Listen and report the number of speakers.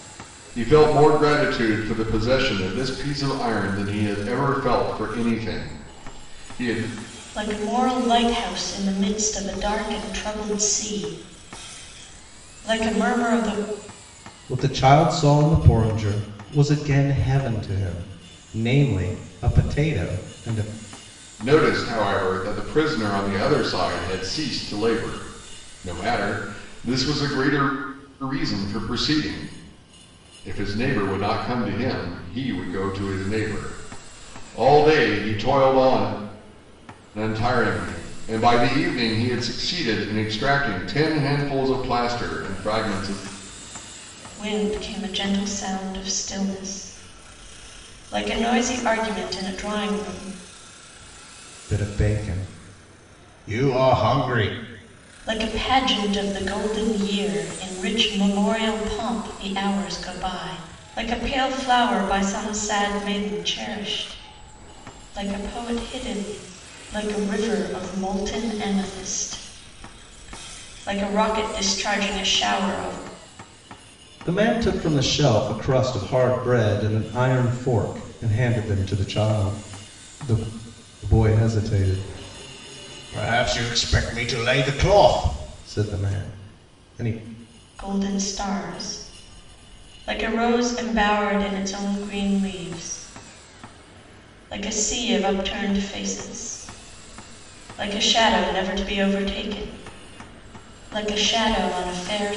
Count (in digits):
3